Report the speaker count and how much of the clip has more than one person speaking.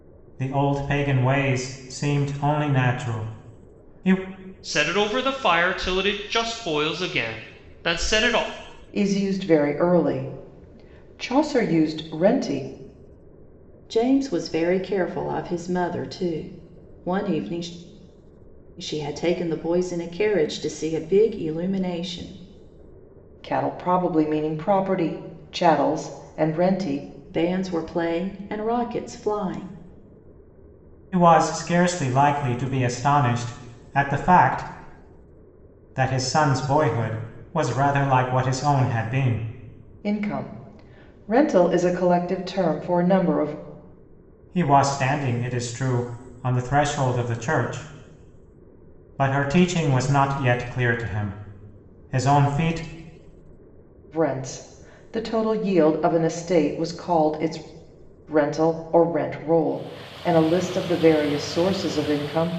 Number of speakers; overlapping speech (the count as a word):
four, no overlap